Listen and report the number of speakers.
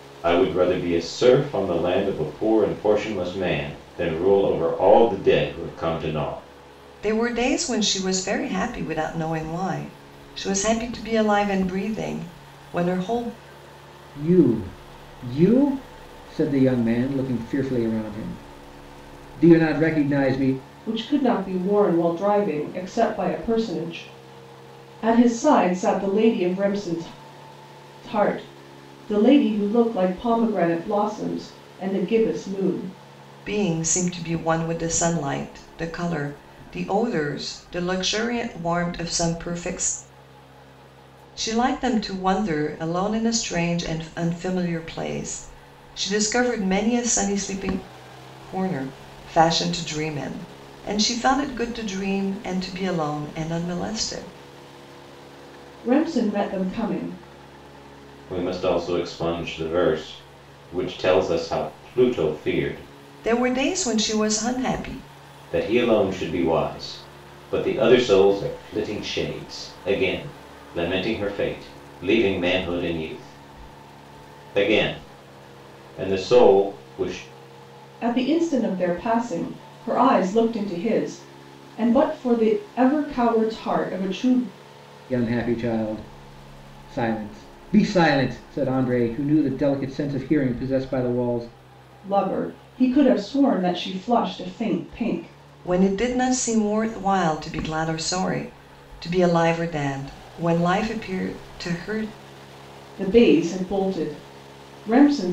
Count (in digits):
4